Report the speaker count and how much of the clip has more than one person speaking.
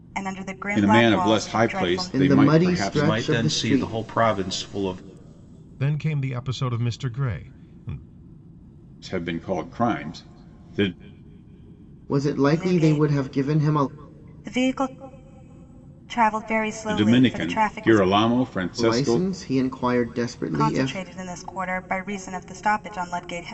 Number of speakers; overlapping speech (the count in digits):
5, about 29%